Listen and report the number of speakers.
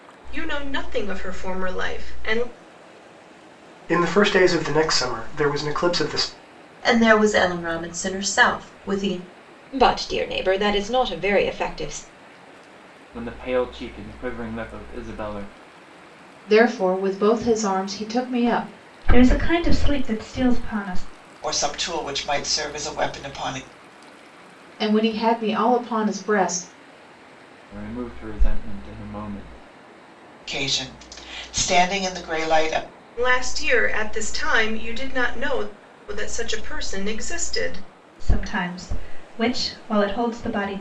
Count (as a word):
eight